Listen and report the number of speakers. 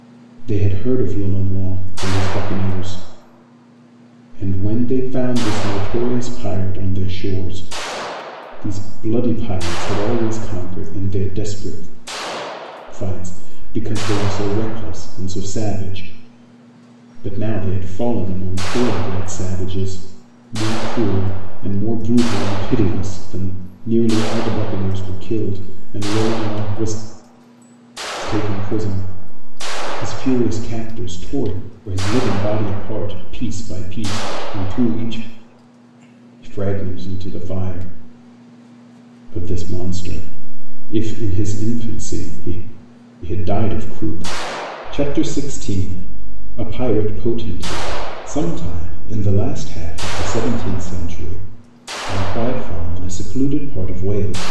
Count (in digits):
1